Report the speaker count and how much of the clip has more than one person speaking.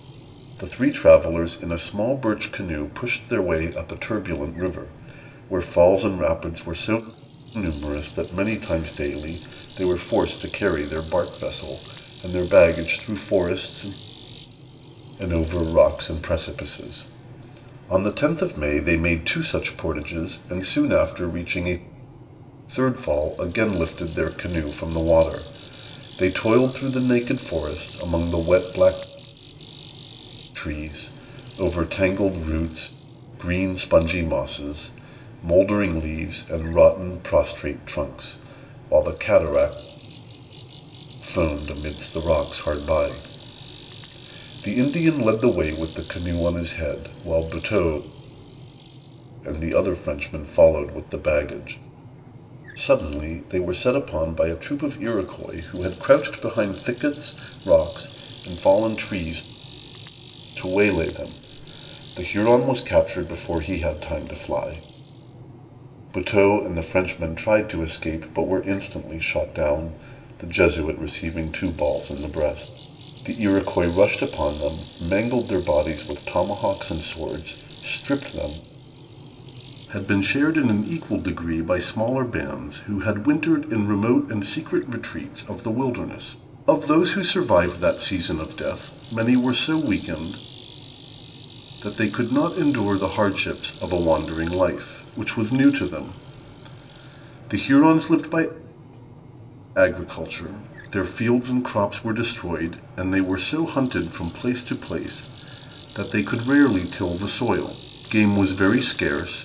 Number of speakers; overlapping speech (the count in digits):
1, no overlap